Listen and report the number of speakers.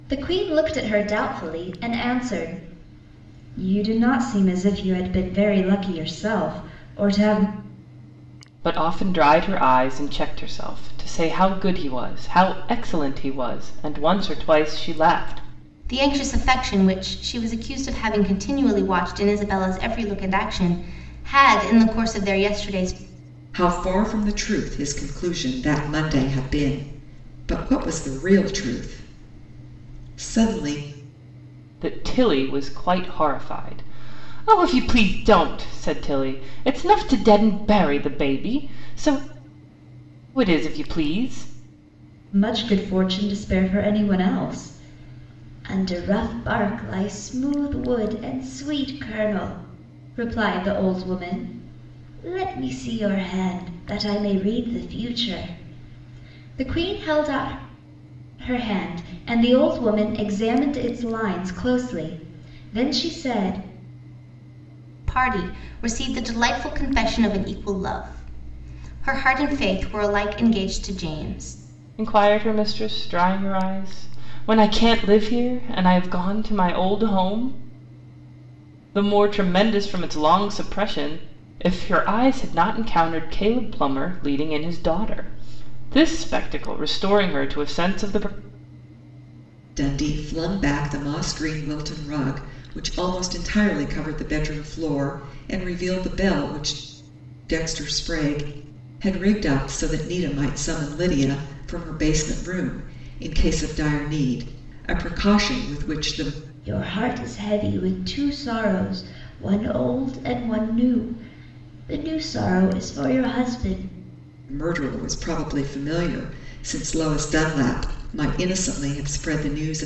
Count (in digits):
4